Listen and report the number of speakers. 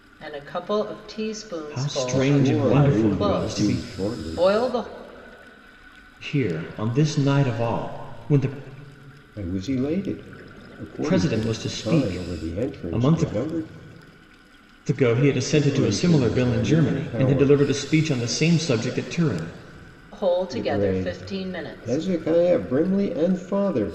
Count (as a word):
three